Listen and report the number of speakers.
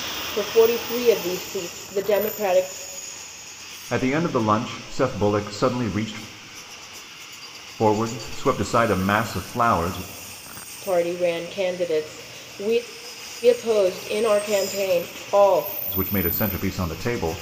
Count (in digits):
2